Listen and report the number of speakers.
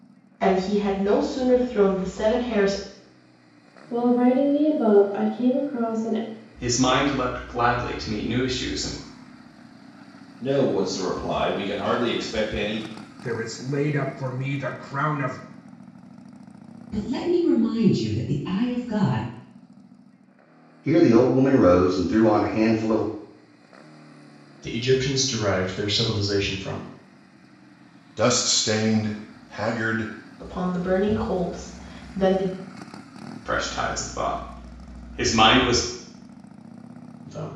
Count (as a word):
nine